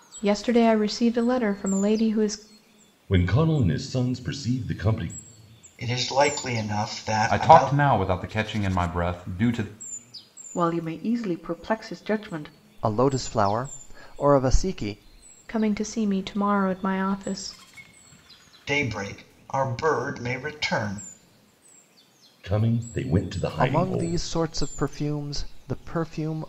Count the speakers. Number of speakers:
6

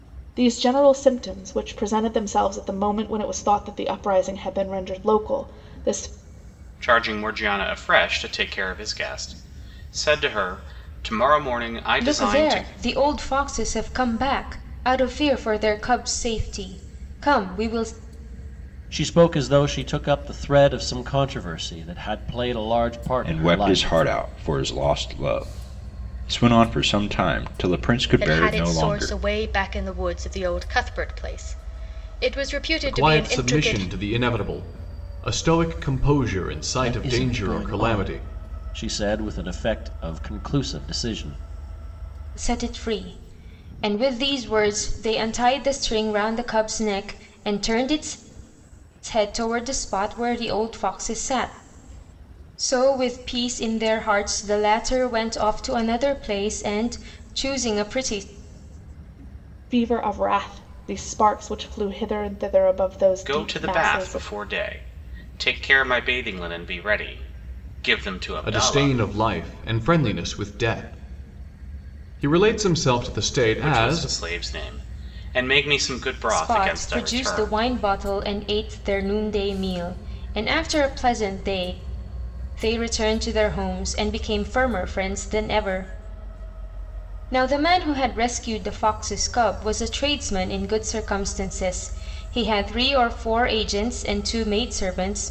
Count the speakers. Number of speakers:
7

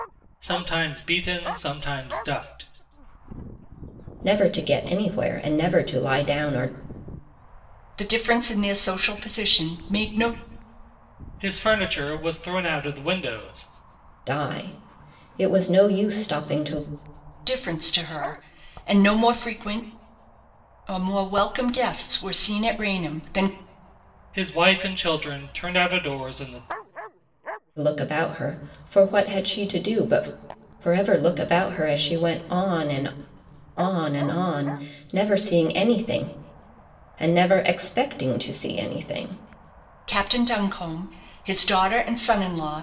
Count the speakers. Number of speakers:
3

